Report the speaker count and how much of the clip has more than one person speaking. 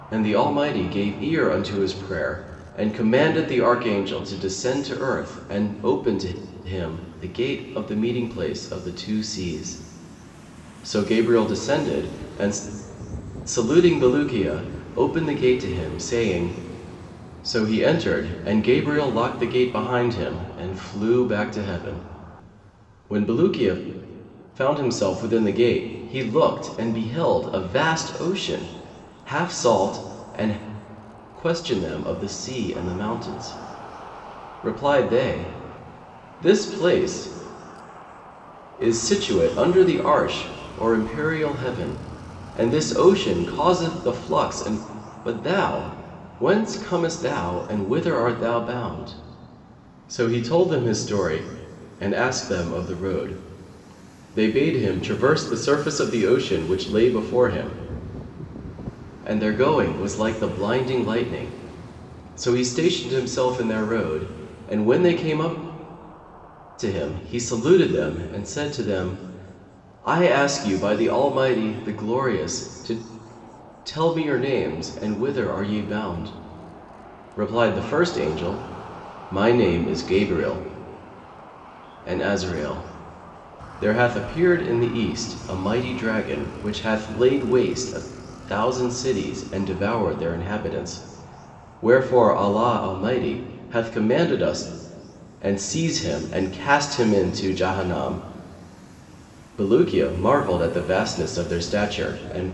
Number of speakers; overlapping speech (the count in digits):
1, no overlap